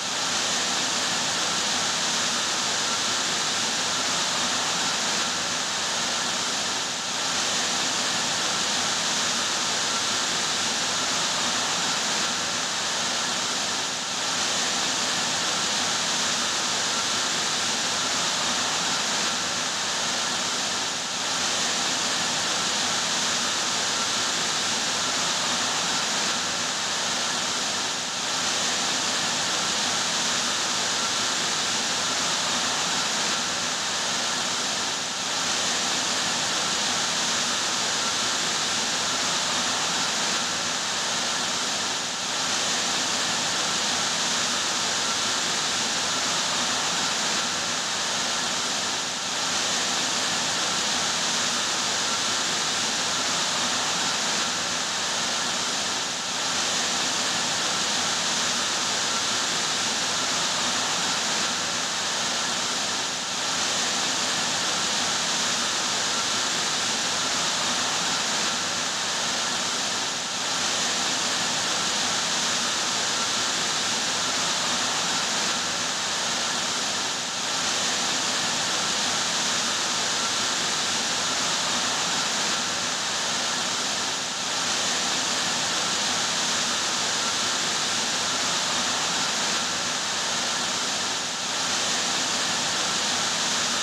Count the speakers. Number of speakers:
zero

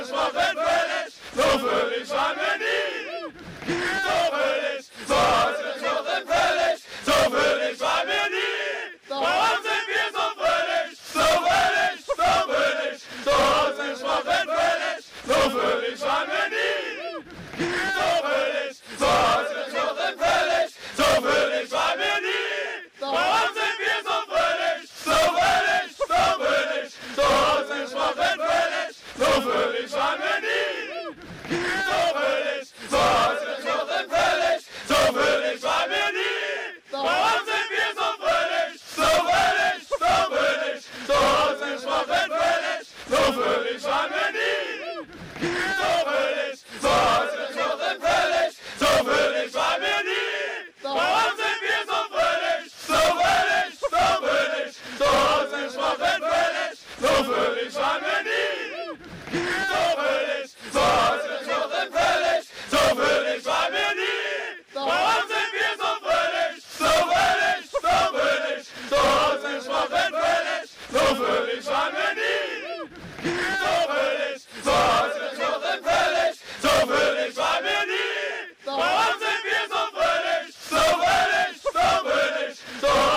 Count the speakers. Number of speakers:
zero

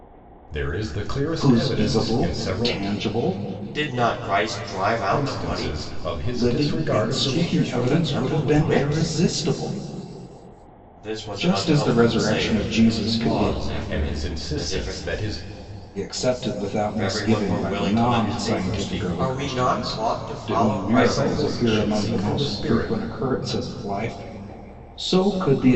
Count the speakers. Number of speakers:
three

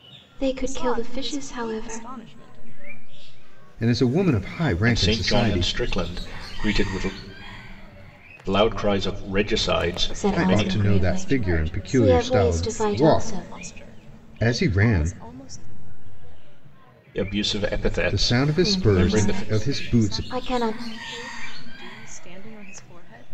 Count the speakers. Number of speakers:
four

